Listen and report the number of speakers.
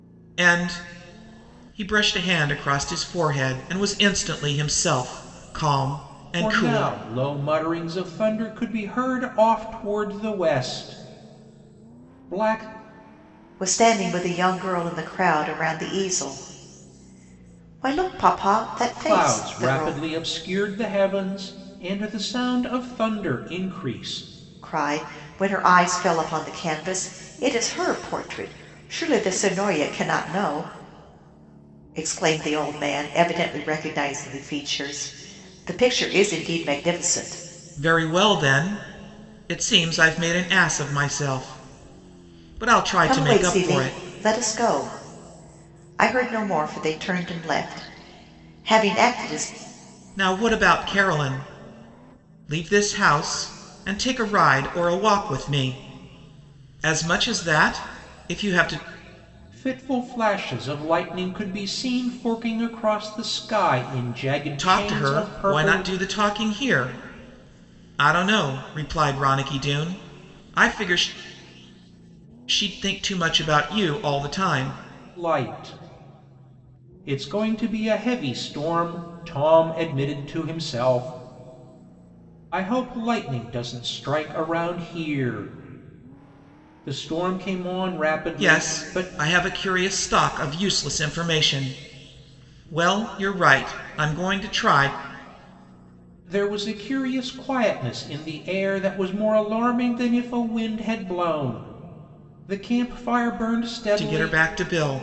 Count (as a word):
three